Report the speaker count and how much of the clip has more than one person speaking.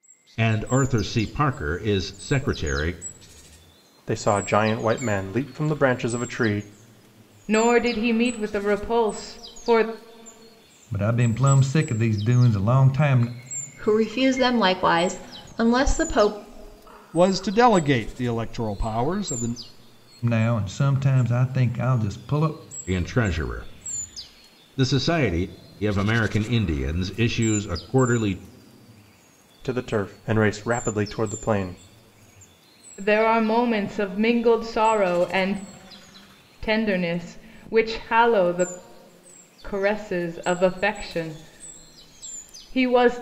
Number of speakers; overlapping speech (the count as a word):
six, no overlap